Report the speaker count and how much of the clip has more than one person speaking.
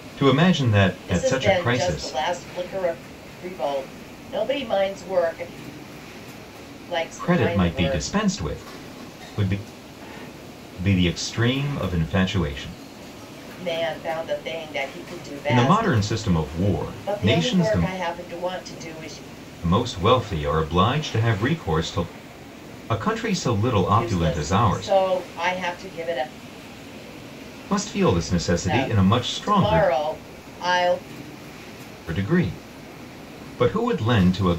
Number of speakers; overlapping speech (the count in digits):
2, about 17%